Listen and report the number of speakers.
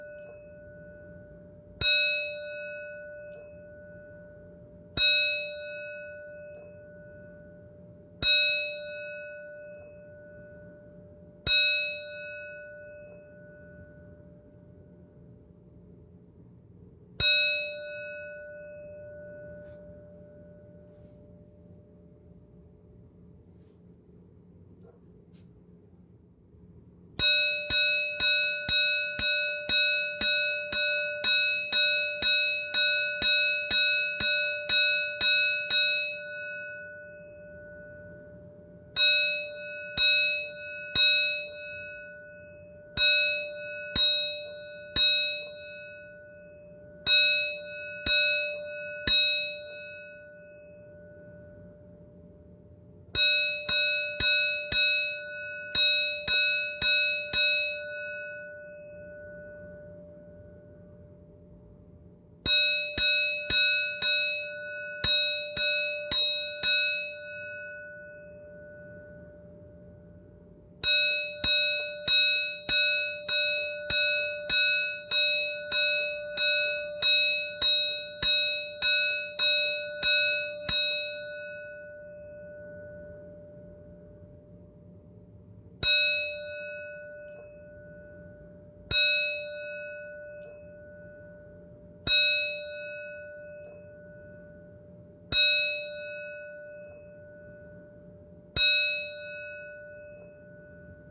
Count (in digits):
0